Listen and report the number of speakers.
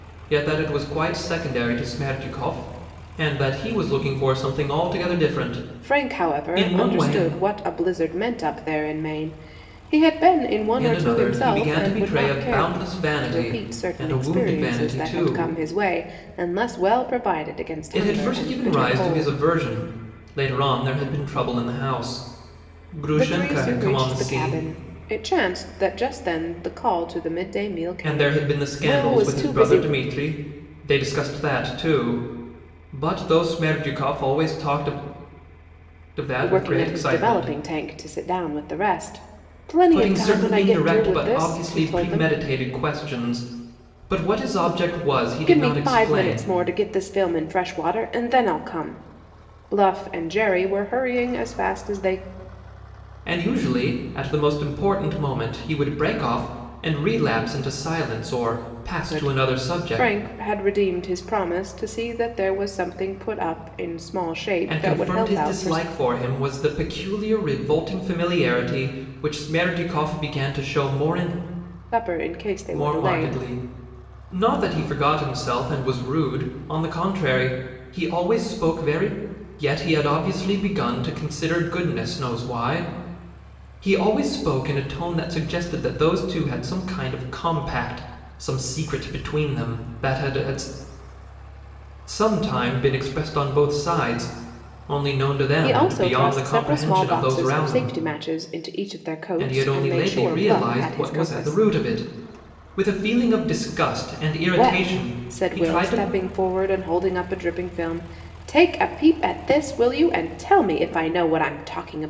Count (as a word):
two